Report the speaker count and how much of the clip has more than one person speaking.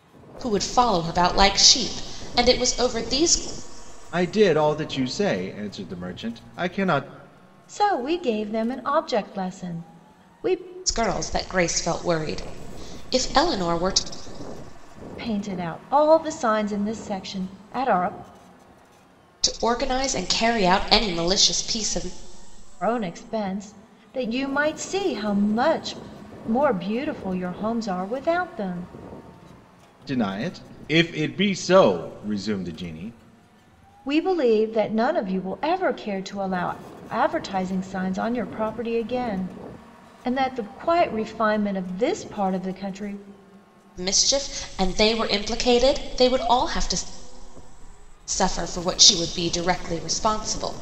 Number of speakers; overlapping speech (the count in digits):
3, no overlap